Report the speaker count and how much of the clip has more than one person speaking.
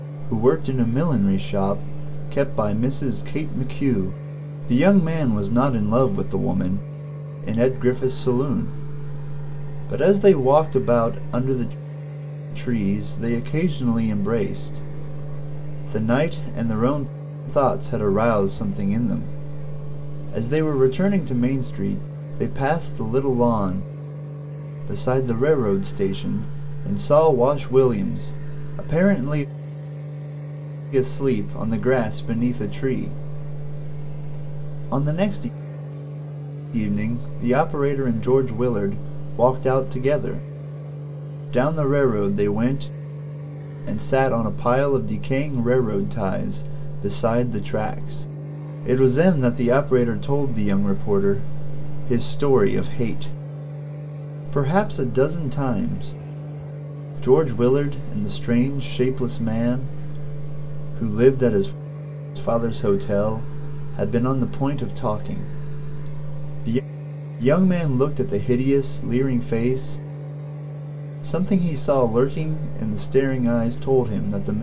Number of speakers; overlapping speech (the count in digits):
1, no overlap